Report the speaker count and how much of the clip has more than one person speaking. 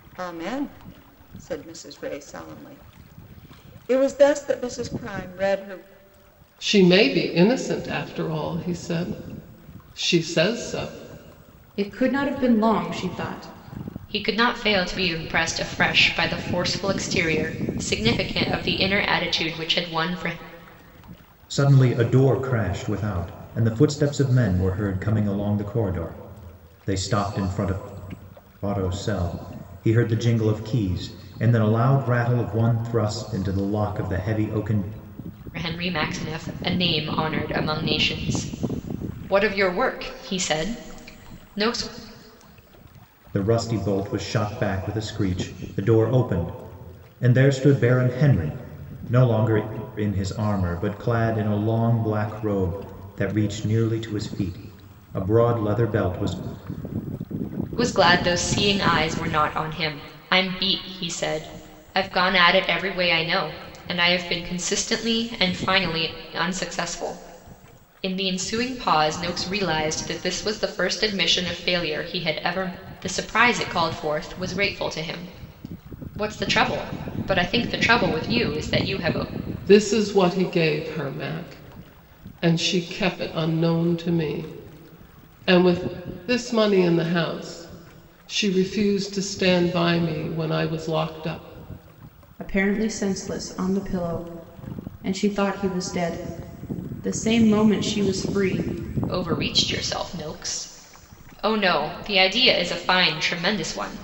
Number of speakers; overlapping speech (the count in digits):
5, no overlap